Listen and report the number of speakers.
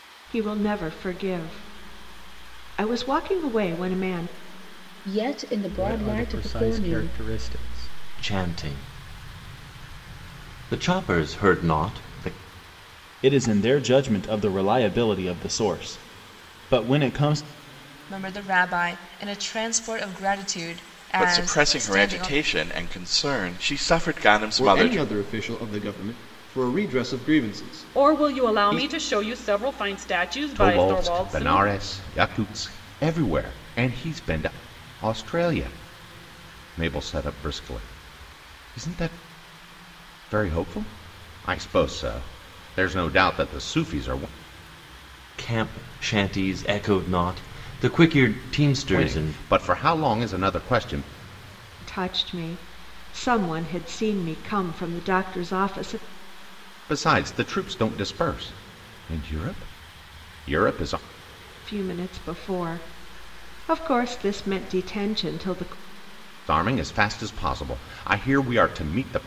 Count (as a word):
ten